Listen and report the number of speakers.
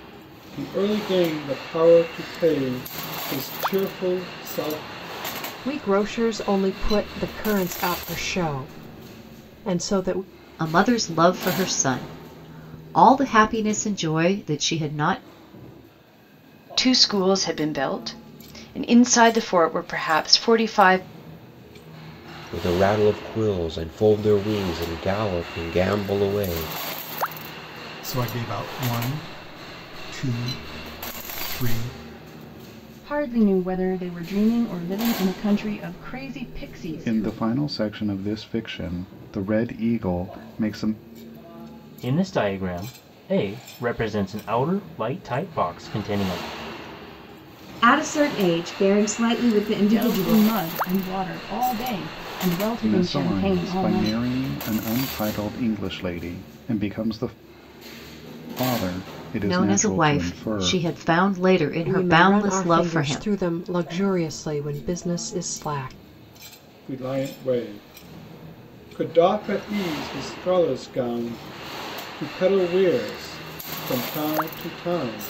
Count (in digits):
10